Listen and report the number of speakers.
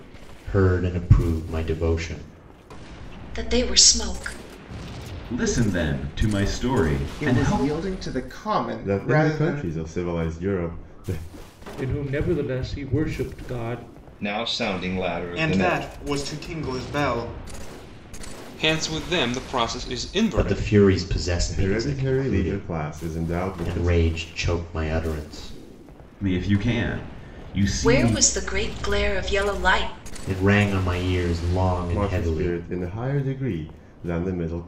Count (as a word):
nine